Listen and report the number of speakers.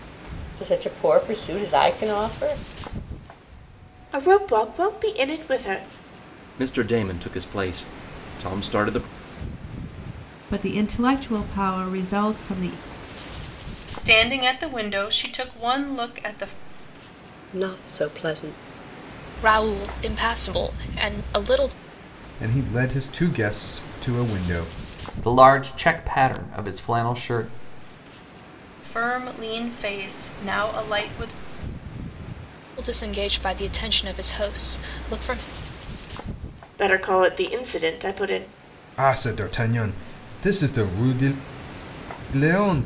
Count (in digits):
9